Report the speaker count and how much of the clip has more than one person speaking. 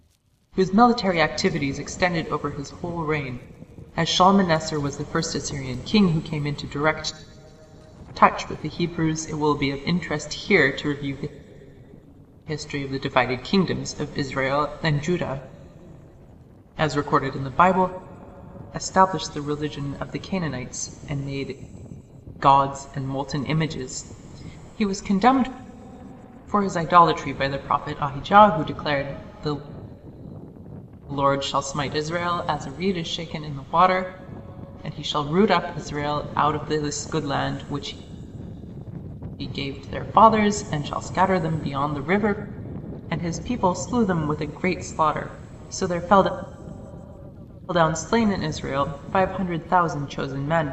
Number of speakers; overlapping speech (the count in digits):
1, no overlap